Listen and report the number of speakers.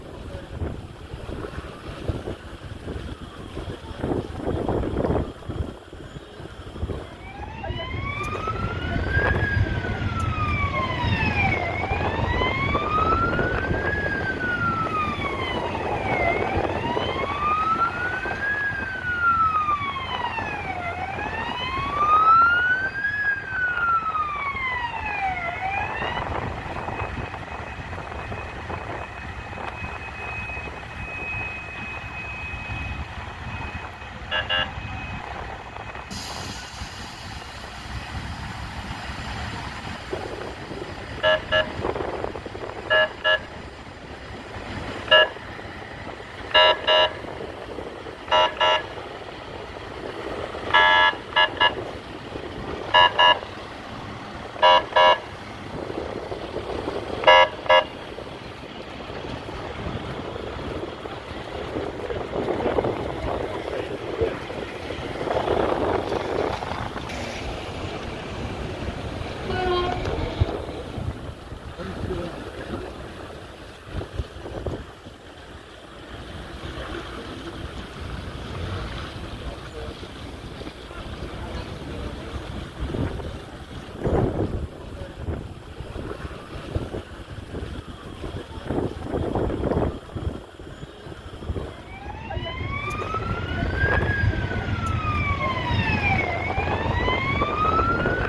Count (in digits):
0